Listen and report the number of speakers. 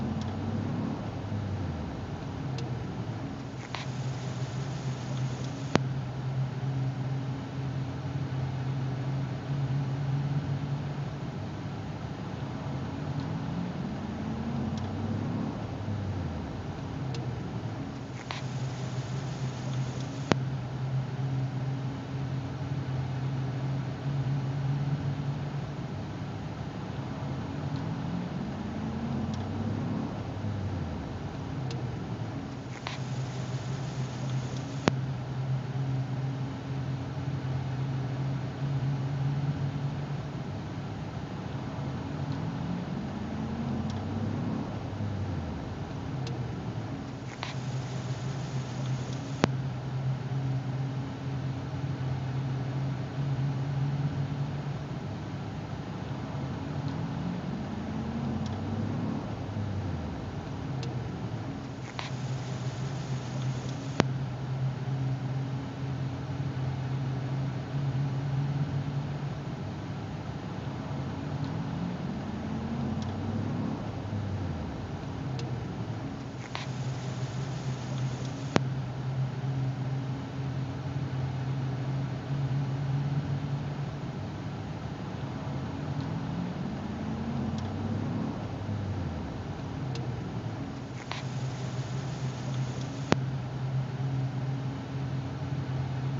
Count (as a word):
zero